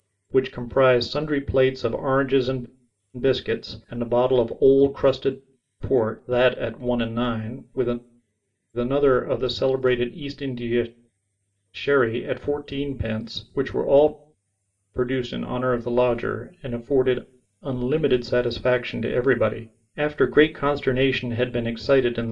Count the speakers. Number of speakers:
1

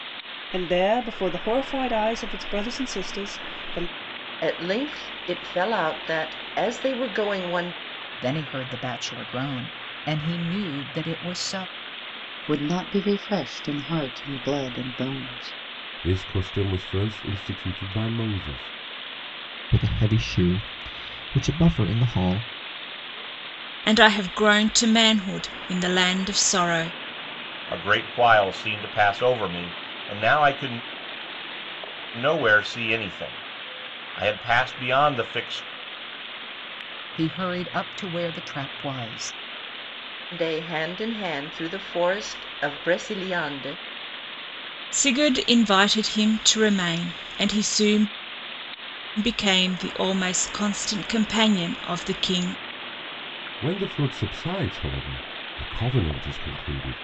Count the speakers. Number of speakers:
8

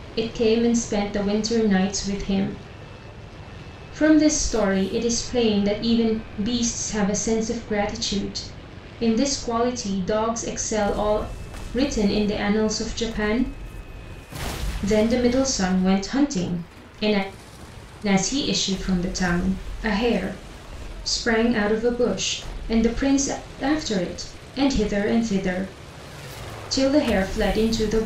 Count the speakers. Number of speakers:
1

